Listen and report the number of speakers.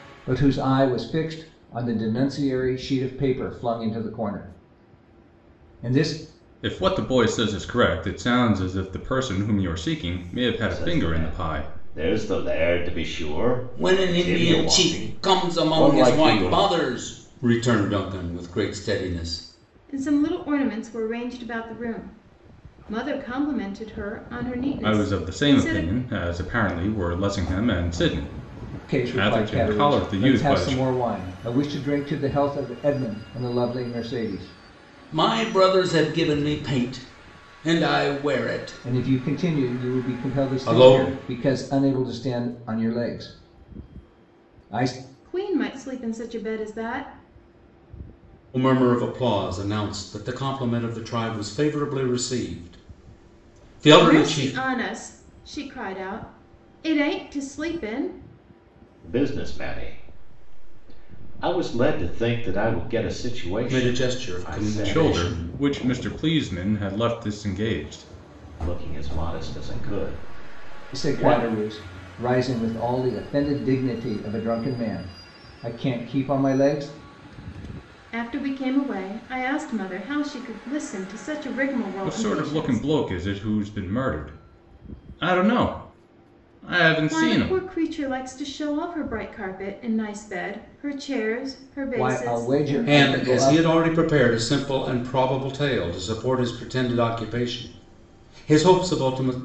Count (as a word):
five